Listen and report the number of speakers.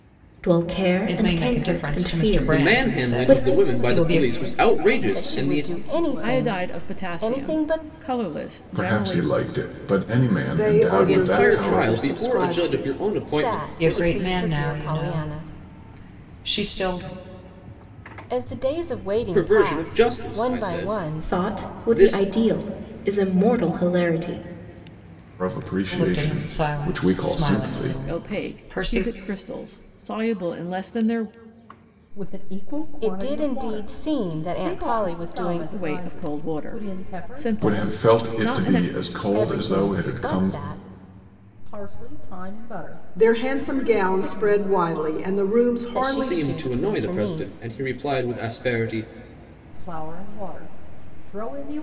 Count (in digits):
8